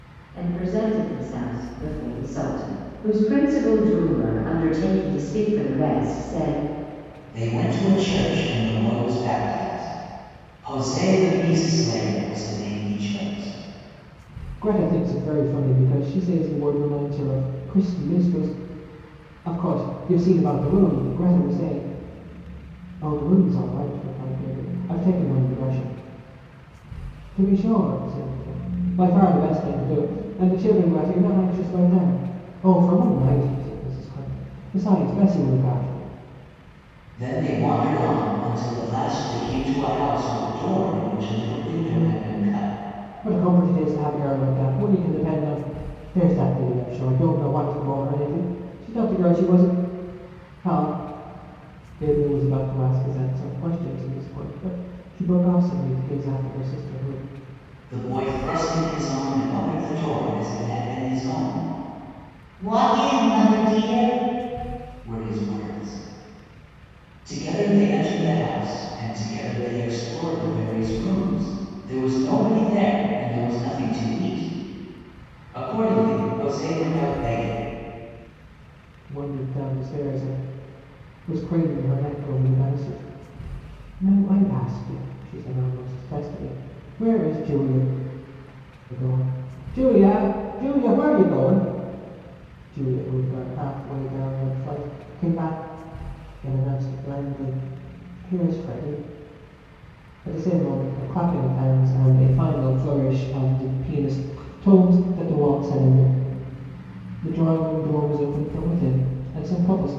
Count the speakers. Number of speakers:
3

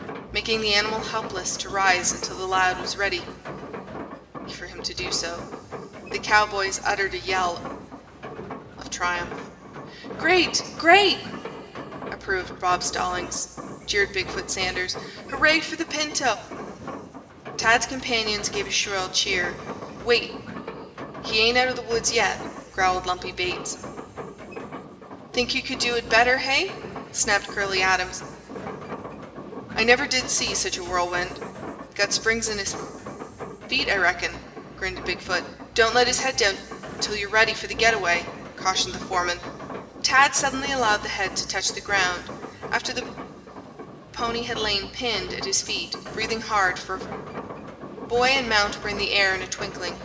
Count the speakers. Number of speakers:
1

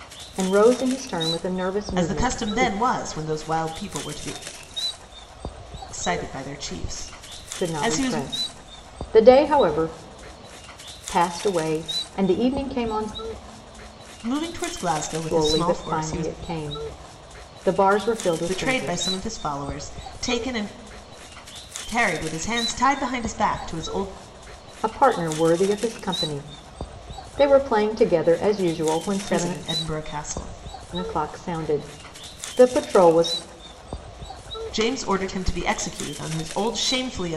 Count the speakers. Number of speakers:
2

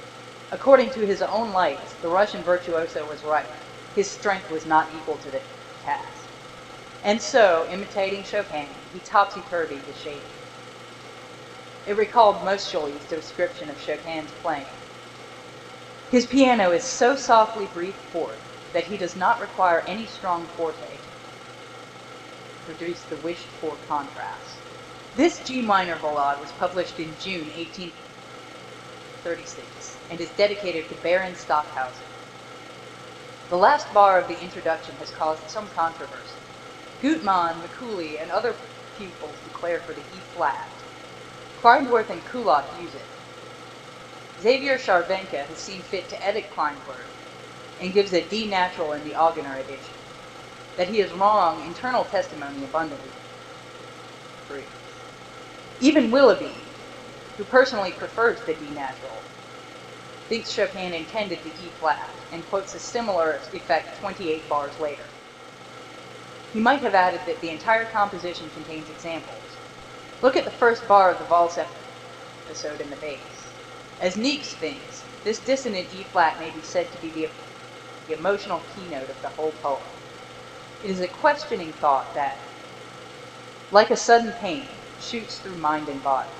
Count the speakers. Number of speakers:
1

